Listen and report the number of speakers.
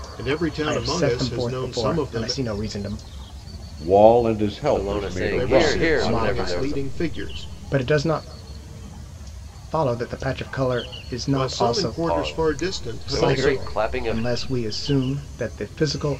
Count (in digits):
4